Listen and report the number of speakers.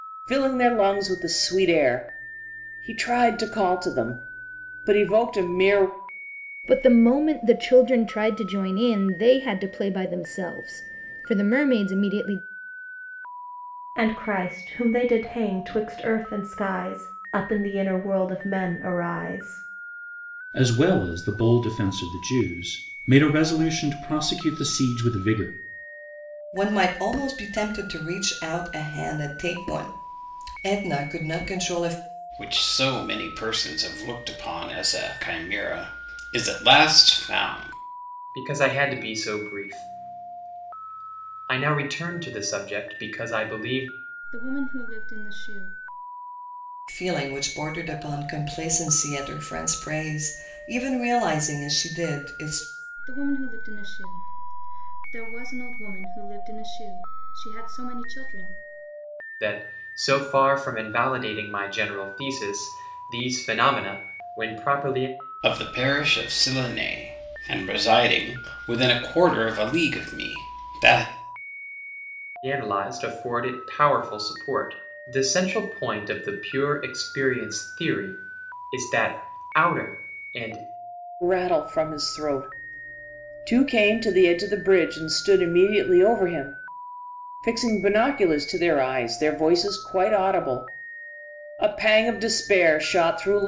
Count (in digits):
8